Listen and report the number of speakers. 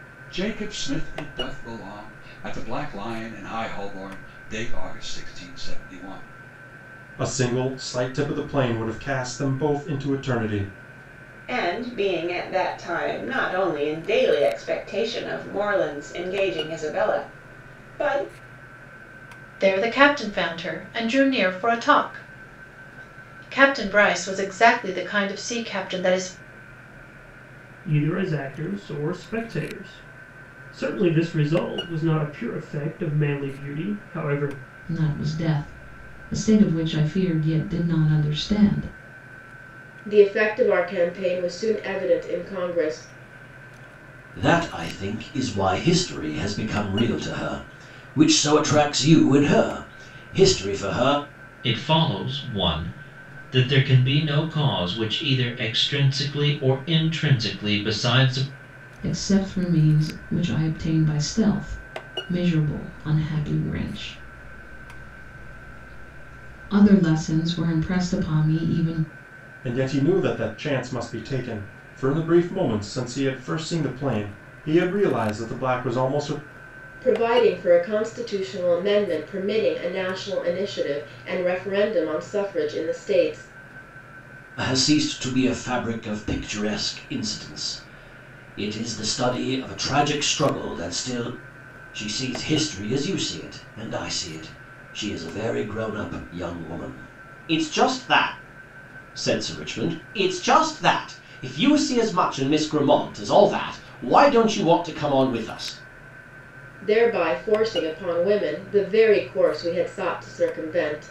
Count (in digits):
9